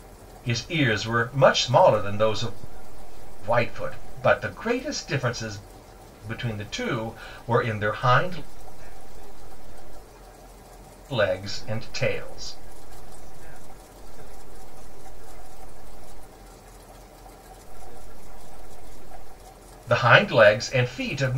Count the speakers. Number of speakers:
2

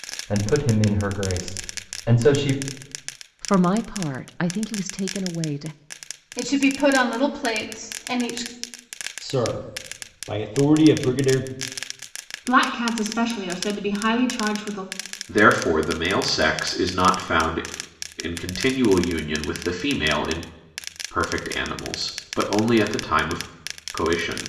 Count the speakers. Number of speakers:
6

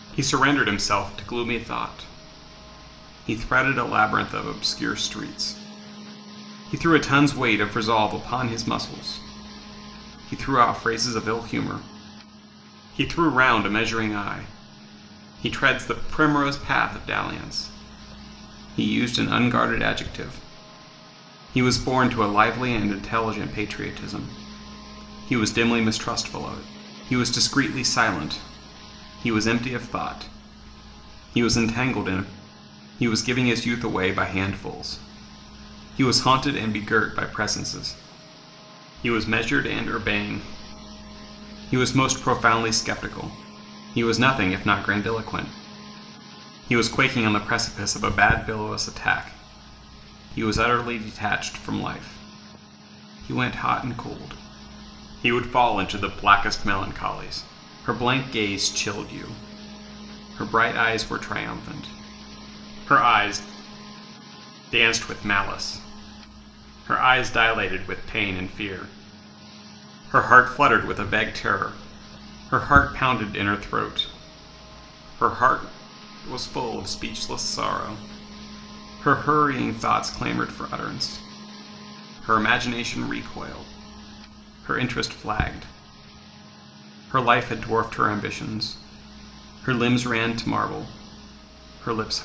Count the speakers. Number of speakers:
1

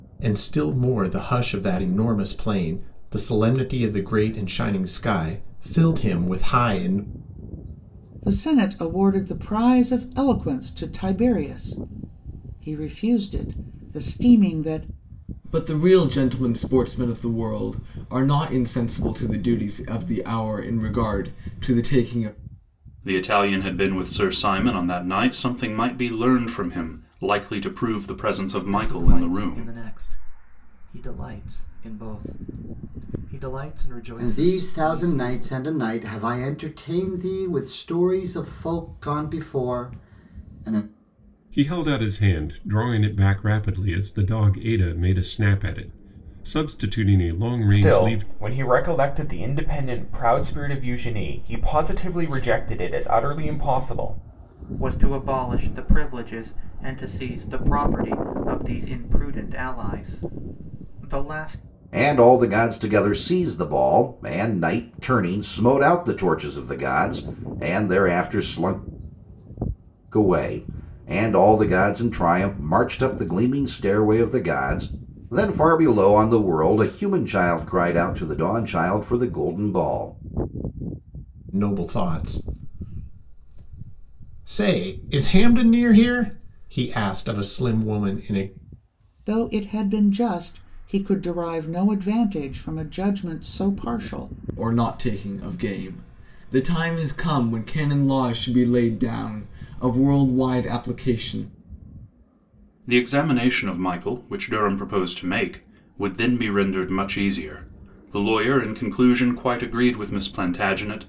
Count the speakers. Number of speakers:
10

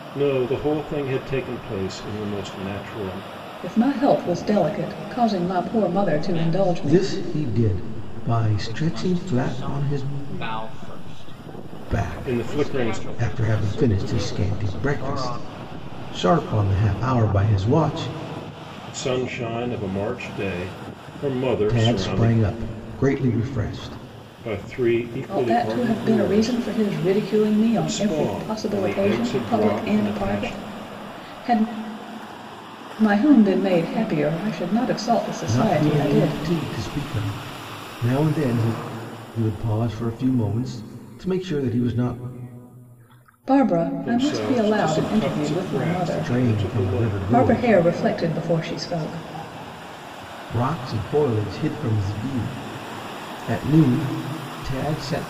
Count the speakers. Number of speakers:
4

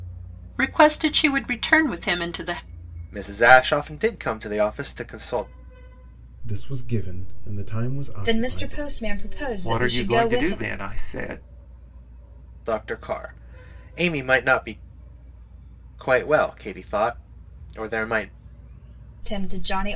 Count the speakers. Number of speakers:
5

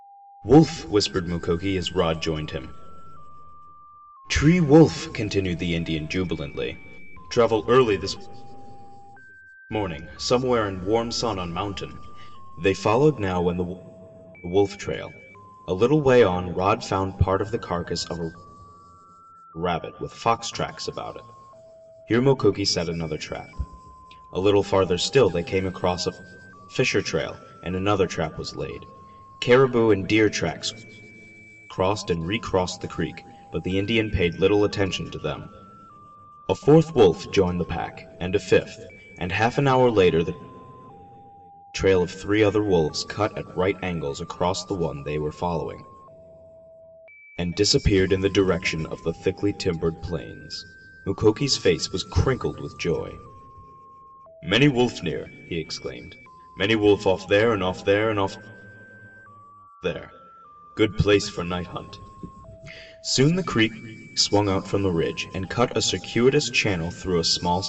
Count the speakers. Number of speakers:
1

